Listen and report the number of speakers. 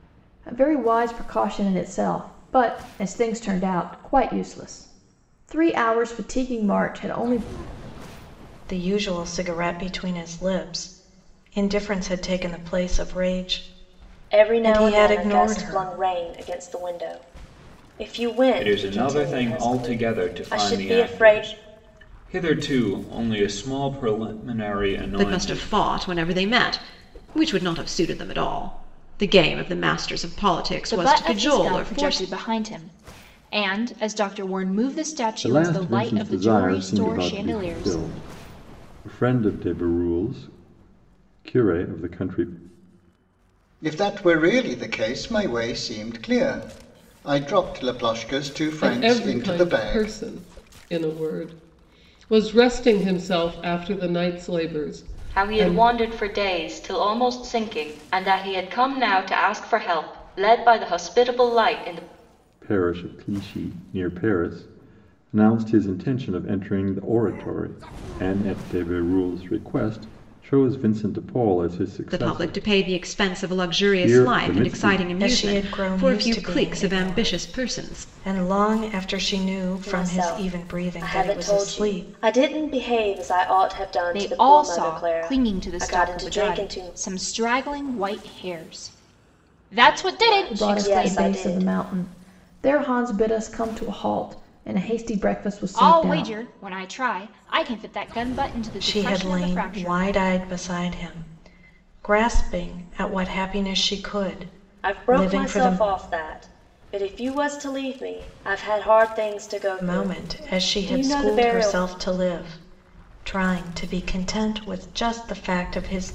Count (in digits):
10